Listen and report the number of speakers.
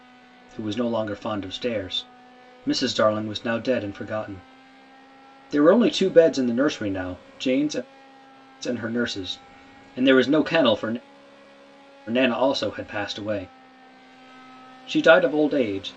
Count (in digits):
1